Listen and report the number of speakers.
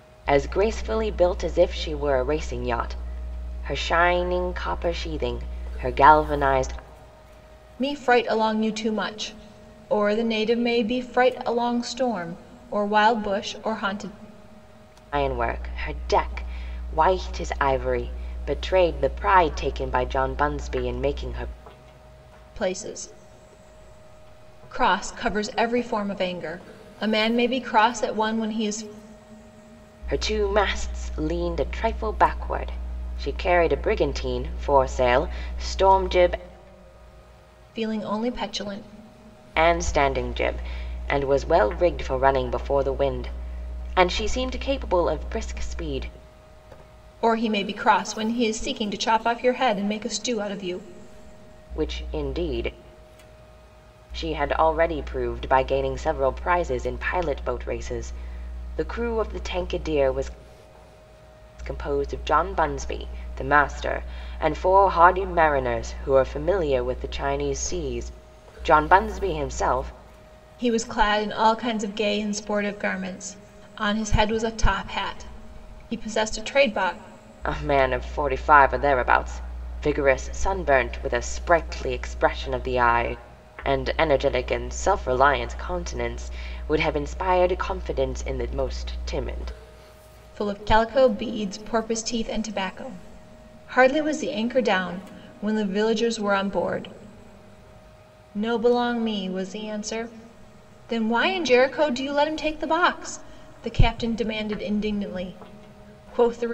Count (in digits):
2